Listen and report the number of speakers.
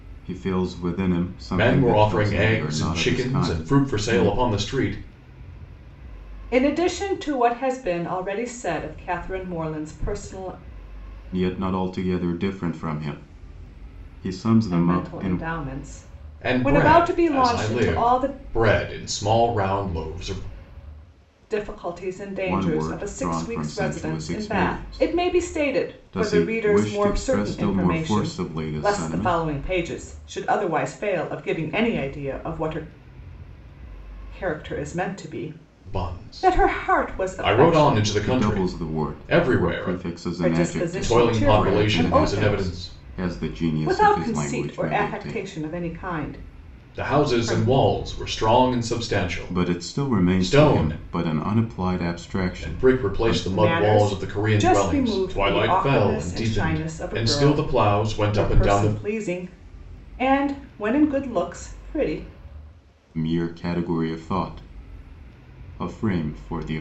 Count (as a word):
three